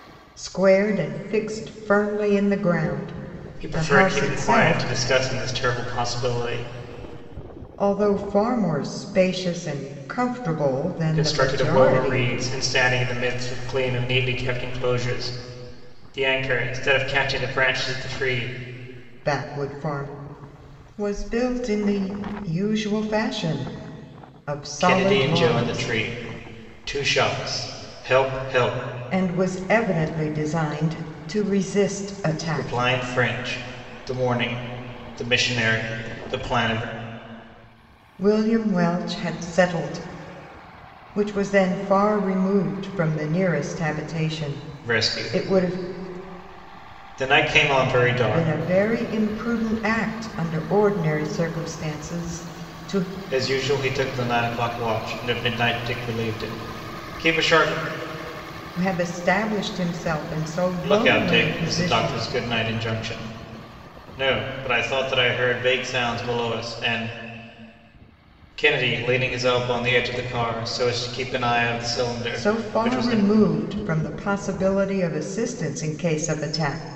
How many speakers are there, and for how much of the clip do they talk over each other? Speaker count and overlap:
two, about 10%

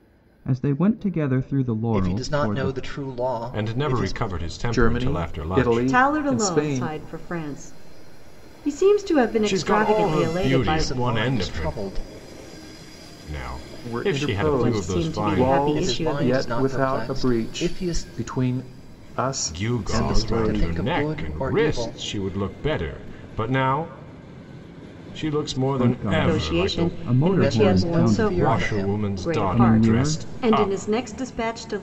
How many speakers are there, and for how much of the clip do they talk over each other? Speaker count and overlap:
five, about 57%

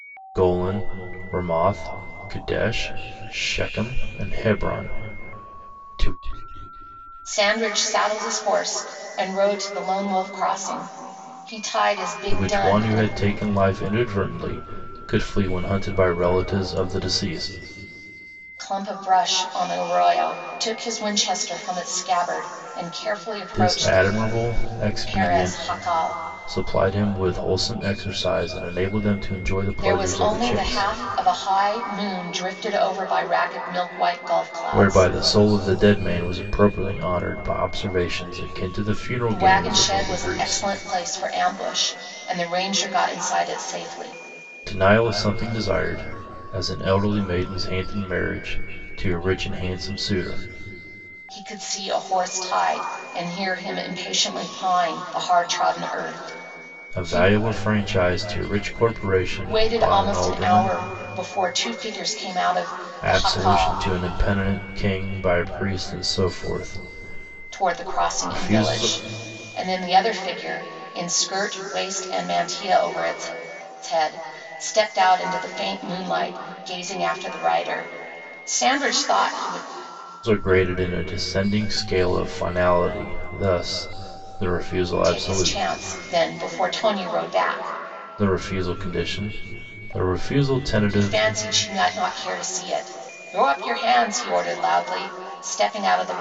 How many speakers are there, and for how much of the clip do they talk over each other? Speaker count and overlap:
two, about 11%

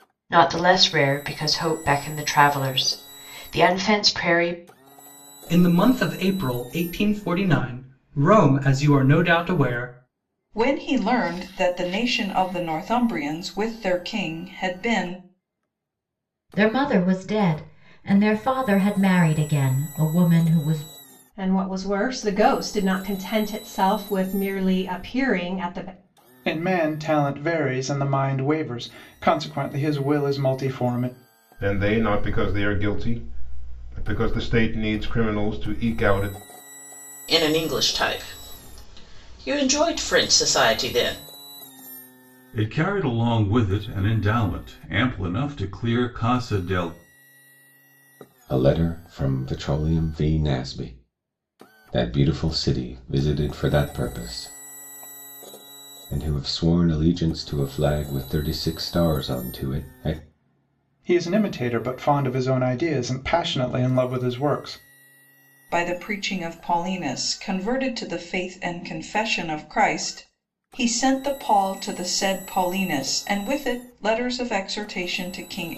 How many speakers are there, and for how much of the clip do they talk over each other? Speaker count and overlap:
ten, no overlap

